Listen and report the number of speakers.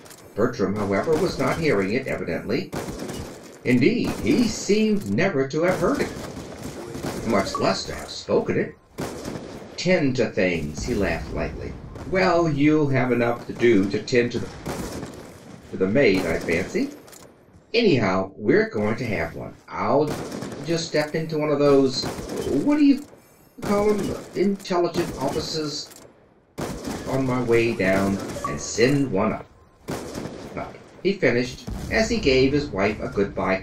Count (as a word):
one